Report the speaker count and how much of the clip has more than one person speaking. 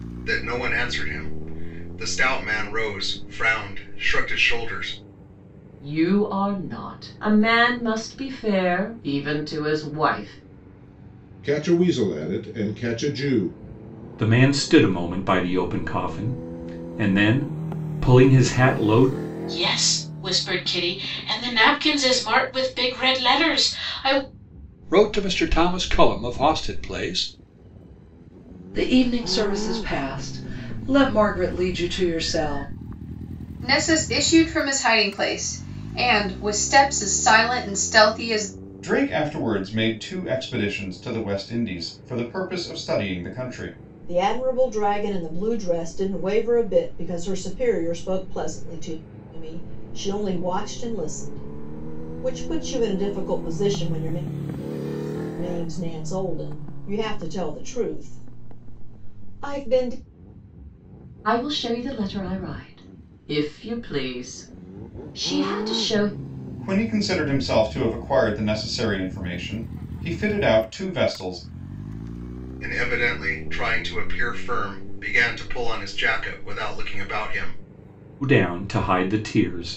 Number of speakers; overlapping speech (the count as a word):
ten, no overlap